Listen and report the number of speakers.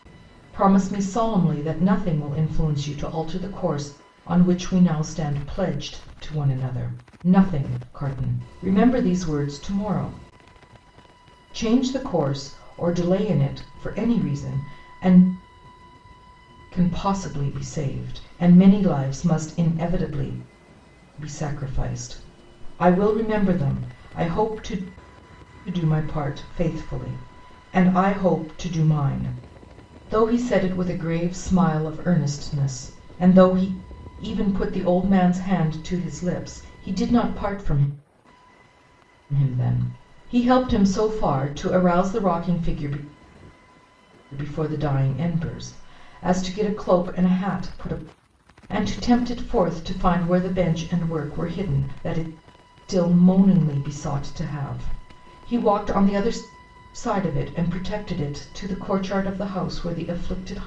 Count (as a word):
one